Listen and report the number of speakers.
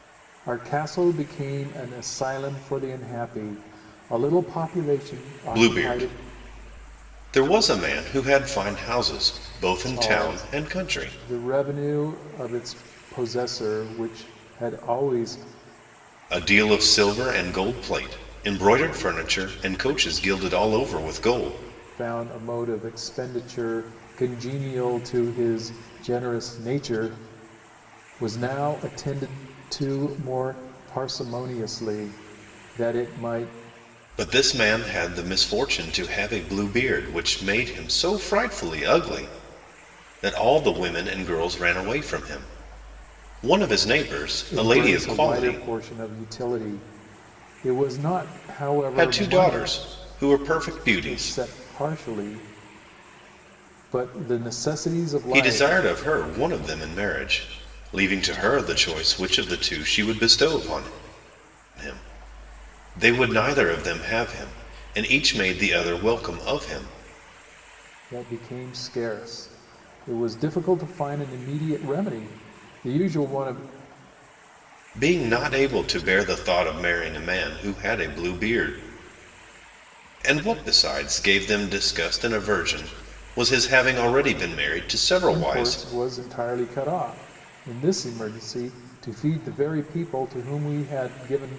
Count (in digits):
2